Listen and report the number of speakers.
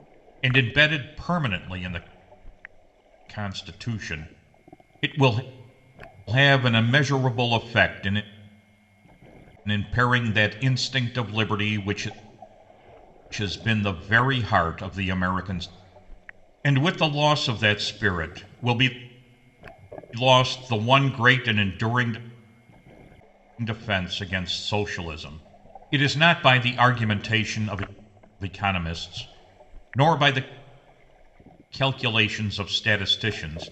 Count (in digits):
1